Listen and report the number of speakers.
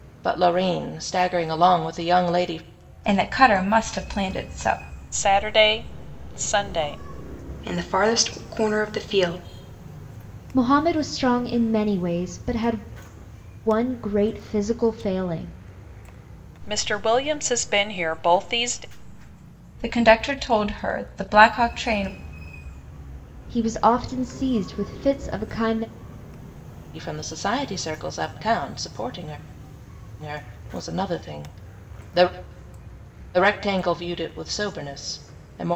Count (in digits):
5